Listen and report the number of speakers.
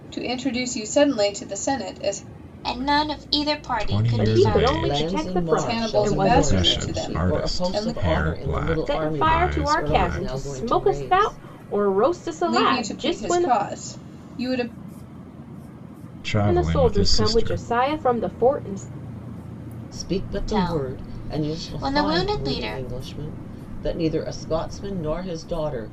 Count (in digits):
5